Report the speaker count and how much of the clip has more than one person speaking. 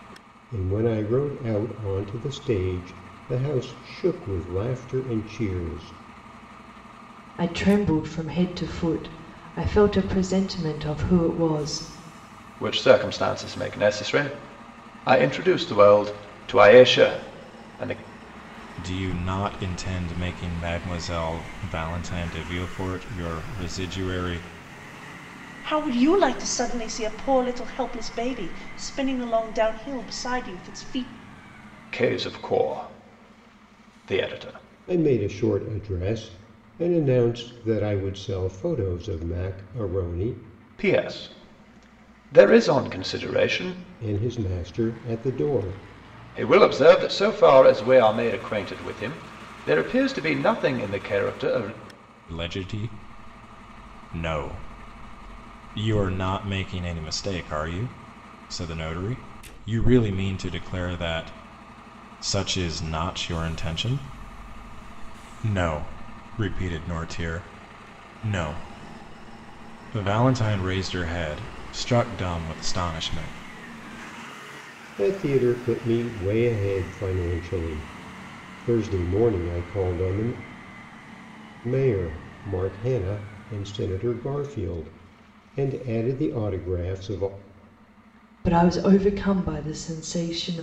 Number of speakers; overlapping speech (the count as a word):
five, no overlap